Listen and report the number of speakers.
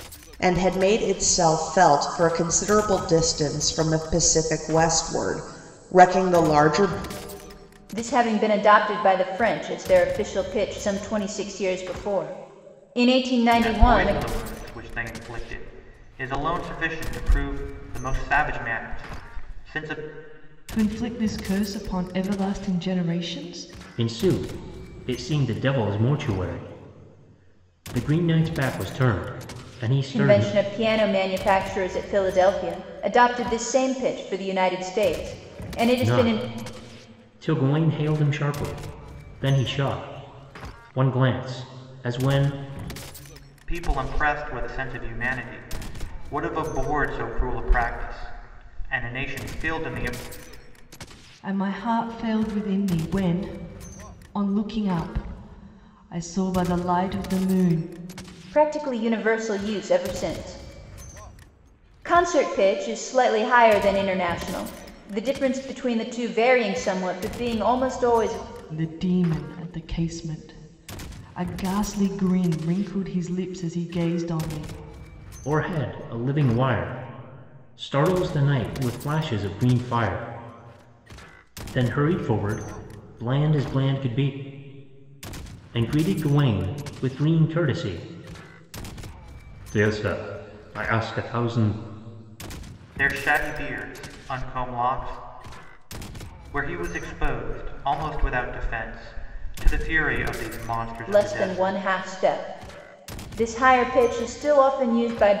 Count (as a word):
five